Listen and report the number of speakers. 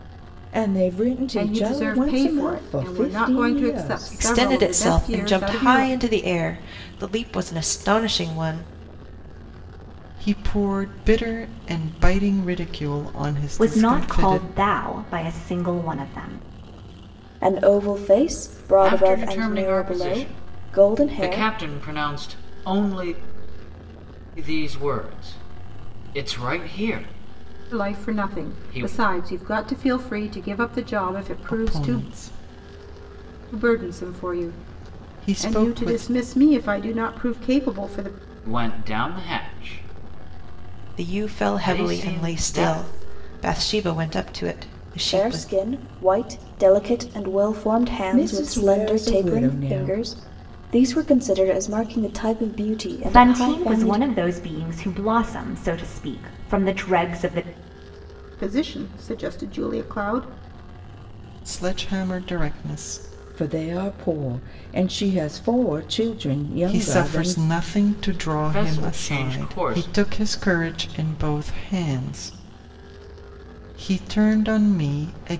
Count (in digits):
7